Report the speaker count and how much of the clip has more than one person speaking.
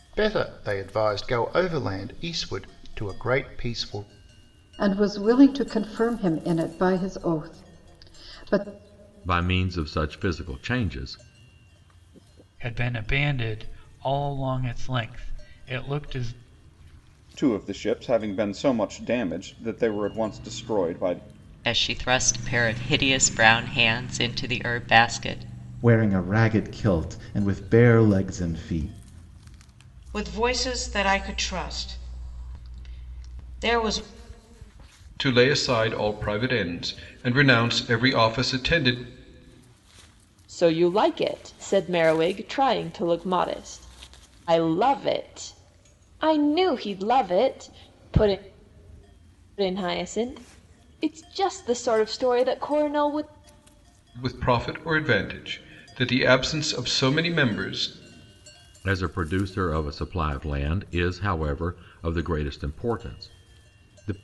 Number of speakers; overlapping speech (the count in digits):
10, no overlap